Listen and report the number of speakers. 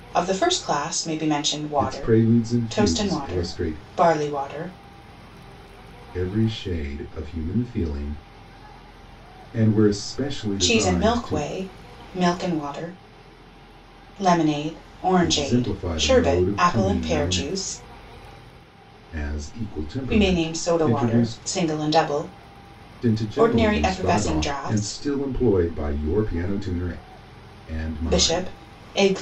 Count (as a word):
two